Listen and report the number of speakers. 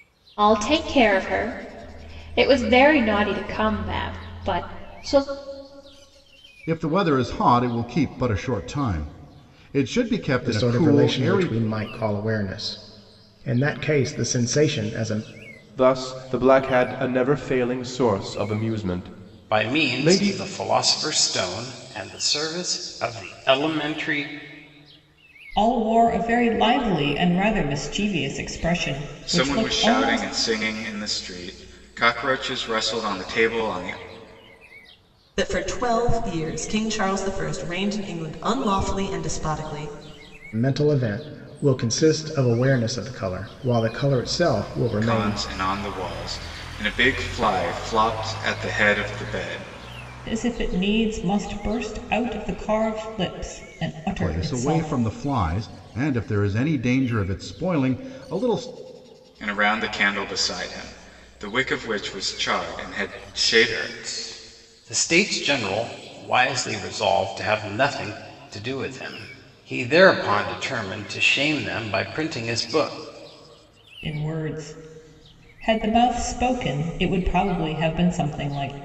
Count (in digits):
8